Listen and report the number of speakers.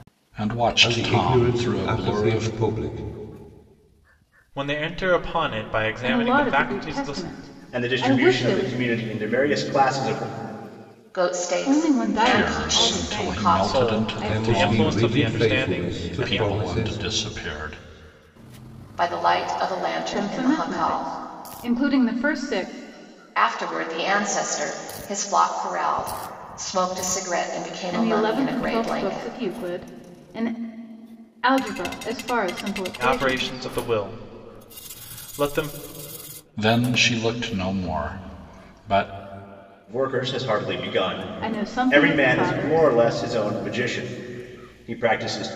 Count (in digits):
6